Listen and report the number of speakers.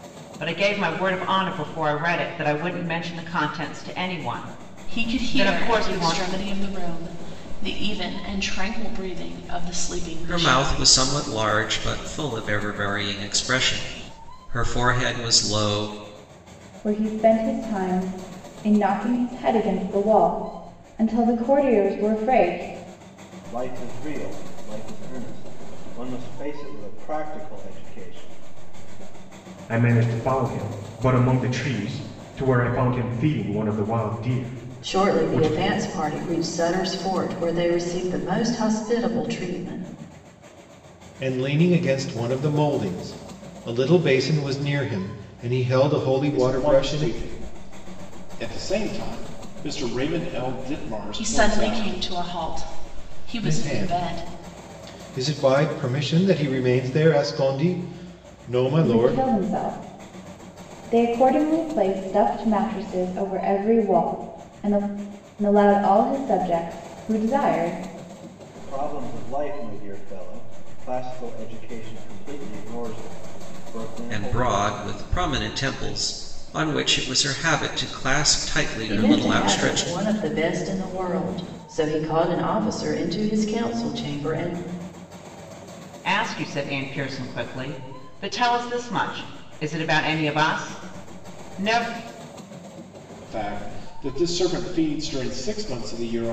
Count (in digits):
9